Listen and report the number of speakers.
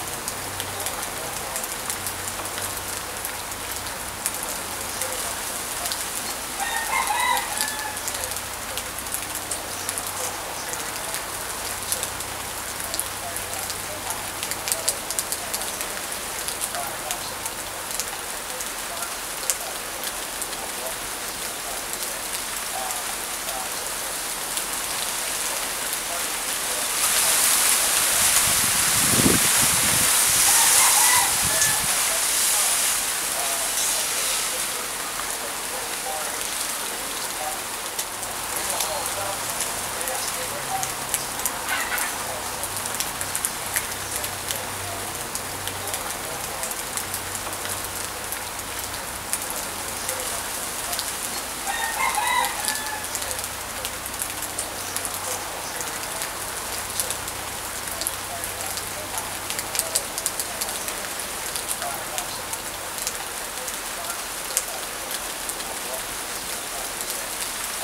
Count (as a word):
zero